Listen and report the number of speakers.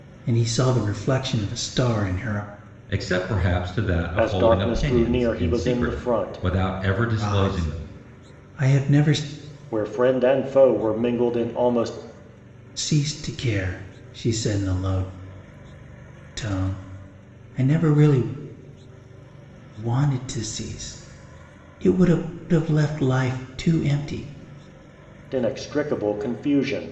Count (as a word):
three